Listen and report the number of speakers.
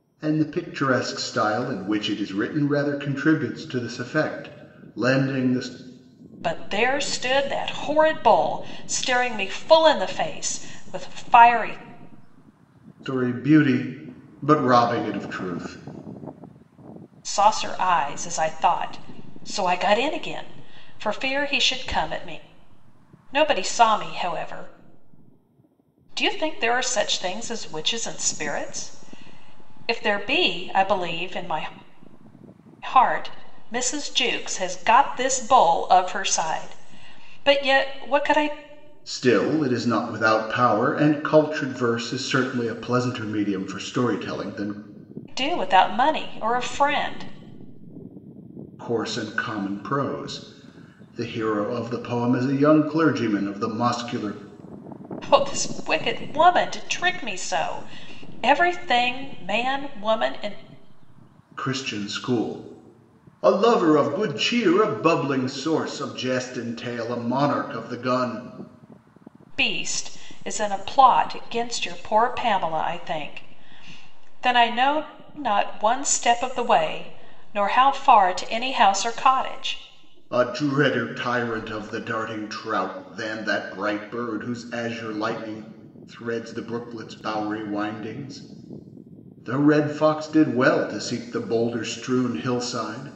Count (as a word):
two